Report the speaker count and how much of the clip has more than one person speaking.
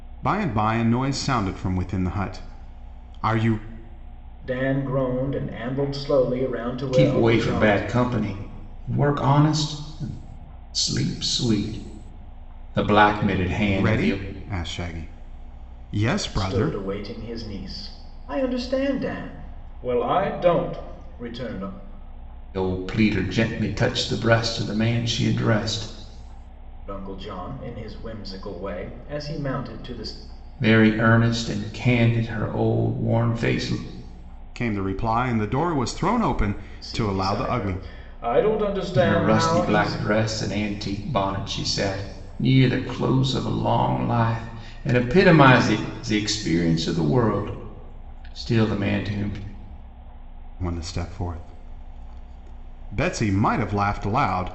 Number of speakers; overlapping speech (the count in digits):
3, about 7%